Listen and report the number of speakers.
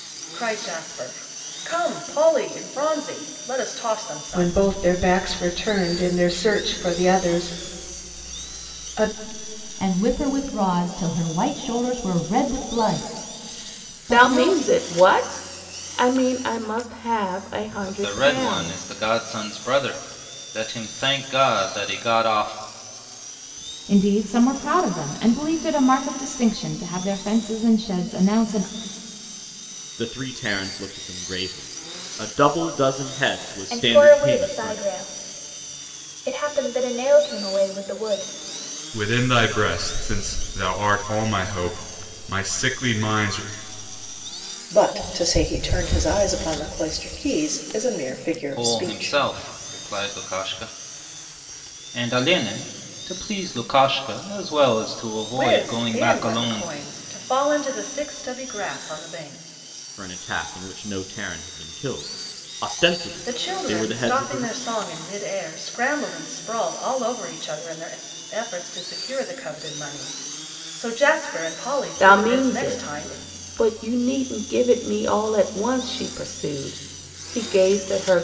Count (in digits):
10